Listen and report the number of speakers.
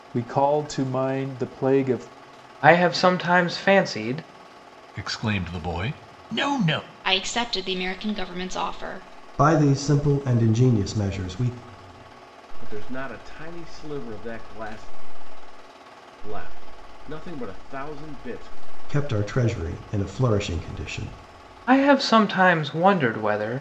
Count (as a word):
six